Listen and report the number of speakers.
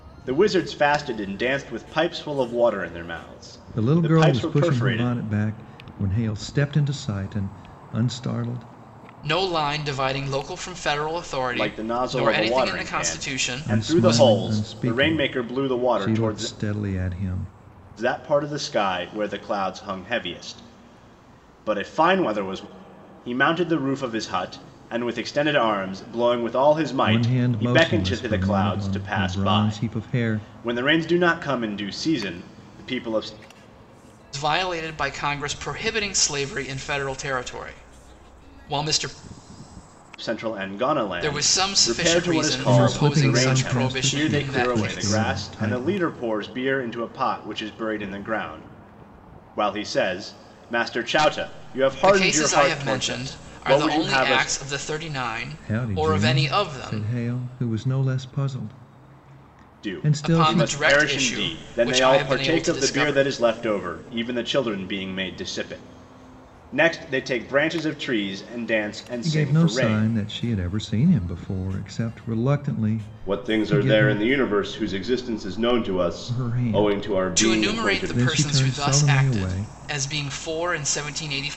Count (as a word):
three